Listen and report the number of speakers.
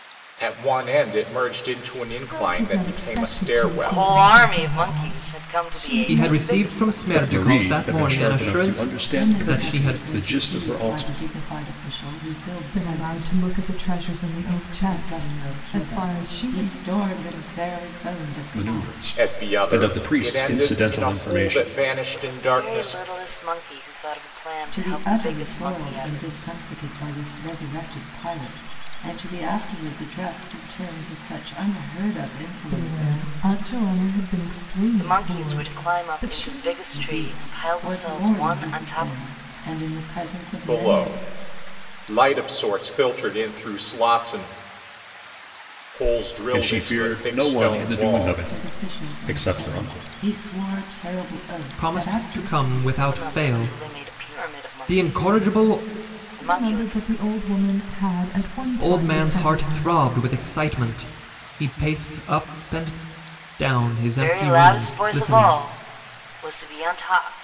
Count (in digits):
6